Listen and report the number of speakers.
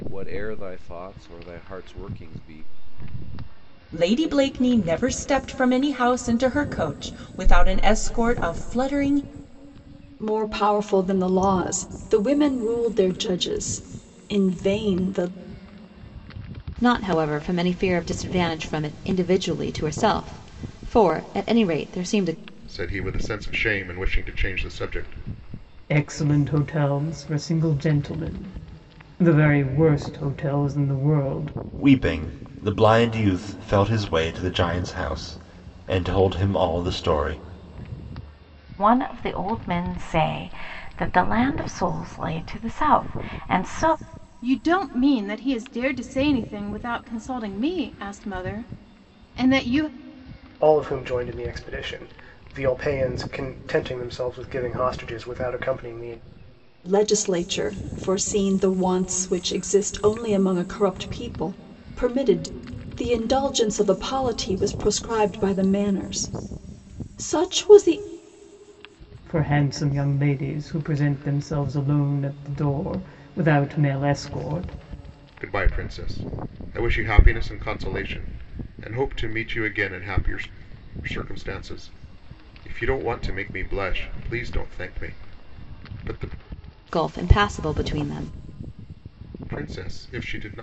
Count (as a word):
ten